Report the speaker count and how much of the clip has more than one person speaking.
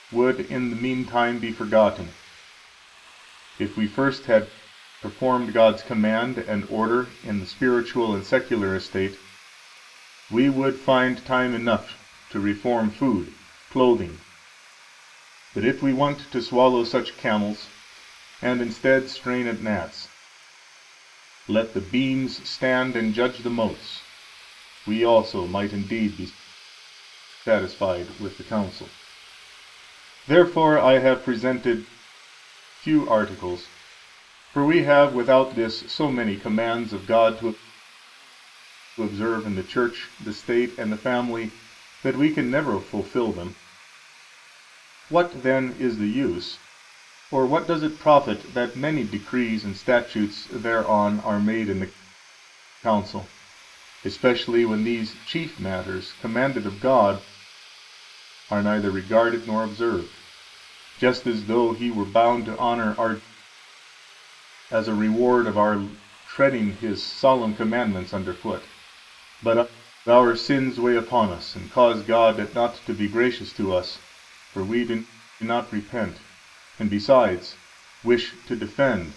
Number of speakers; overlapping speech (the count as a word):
one, no overlap